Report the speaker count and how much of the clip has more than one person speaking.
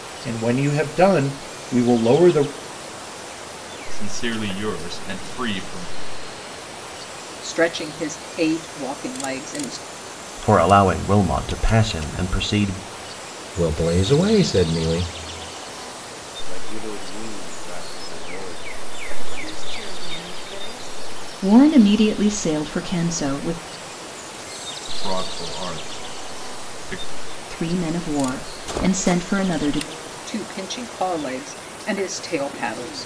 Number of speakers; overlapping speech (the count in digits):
8, no overlap